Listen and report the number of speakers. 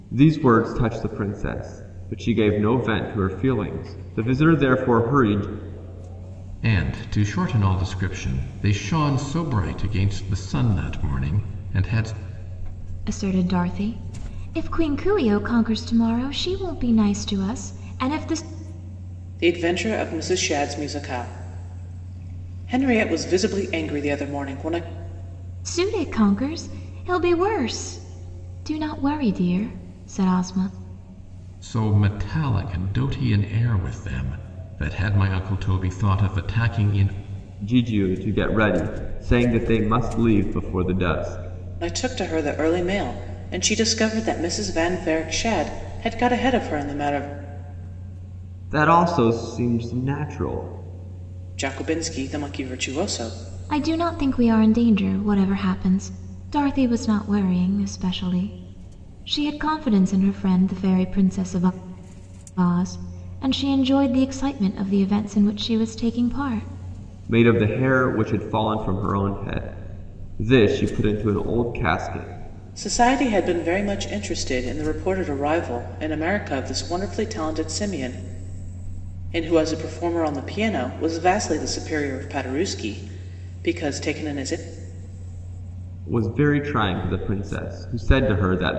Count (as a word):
four